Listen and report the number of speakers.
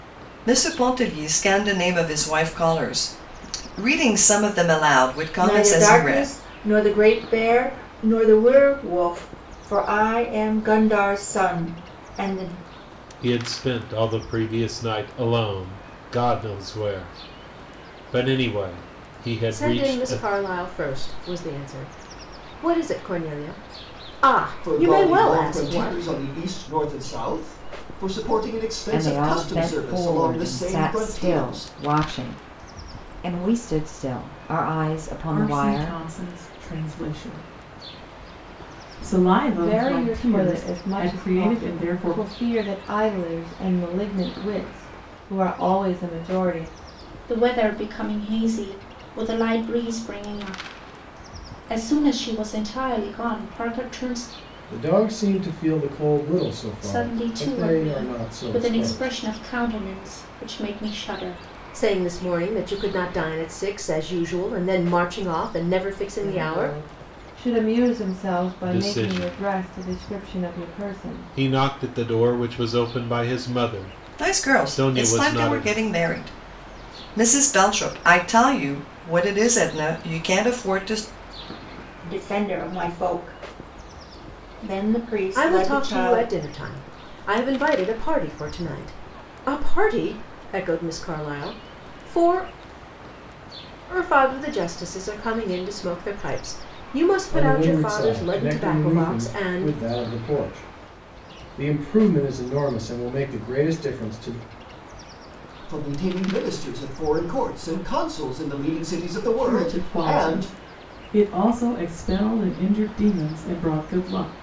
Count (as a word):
ten